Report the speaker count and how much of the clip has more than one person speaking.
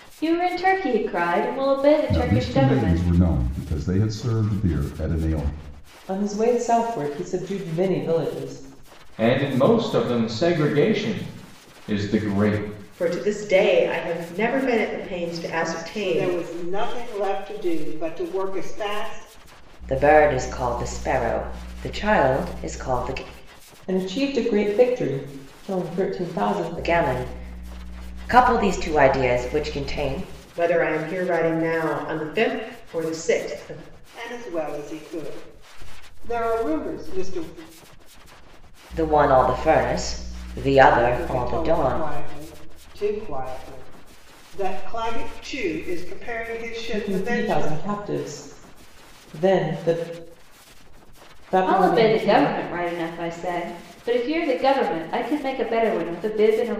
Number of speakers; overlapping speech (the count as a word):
seven, about 8%